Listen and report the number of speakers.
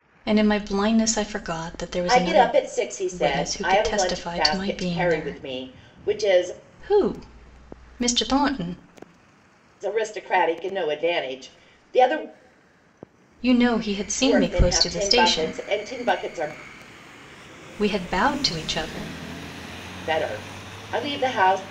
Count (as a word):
two